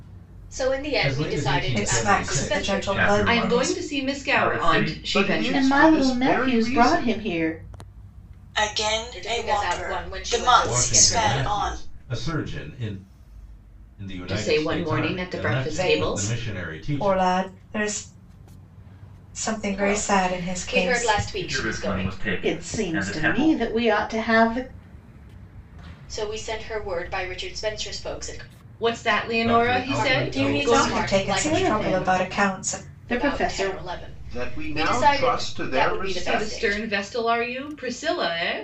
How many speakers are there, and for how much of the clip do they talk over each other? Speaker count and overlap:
eight, about 56%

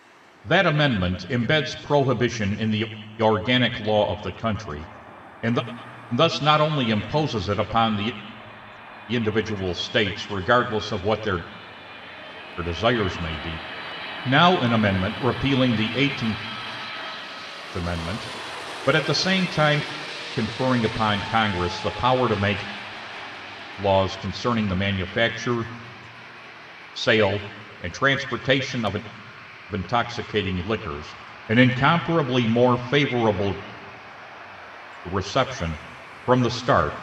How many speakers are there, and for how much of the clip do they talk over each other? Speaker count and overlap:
one, no overlap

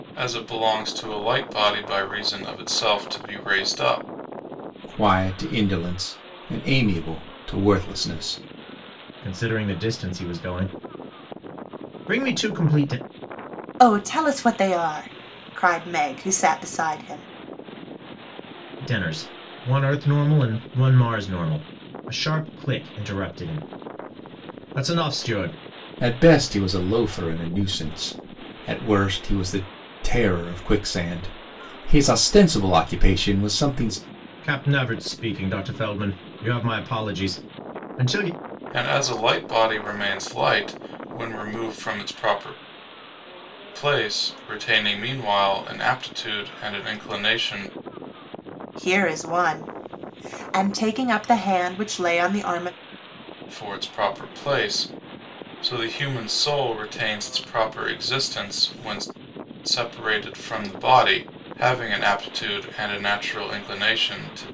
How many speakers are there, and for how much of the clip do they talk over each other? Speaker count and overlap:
four, no overlap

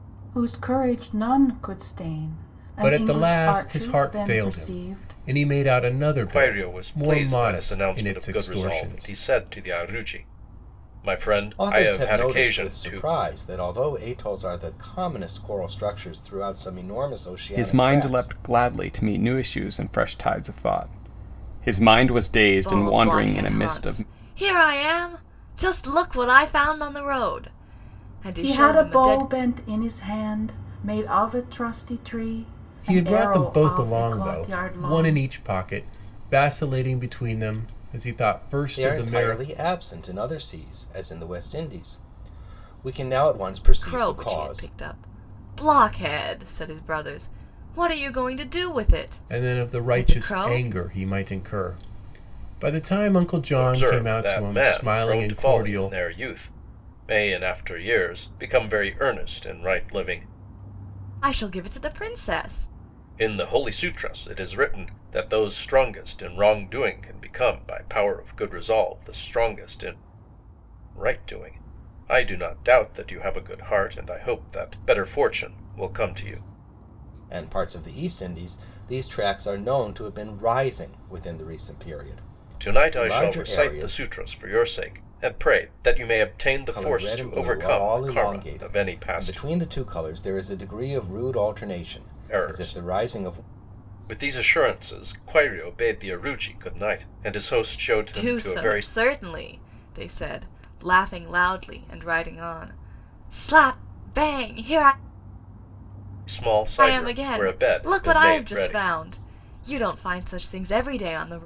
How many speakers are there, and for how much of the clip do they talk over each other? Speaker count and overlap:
six, about 24%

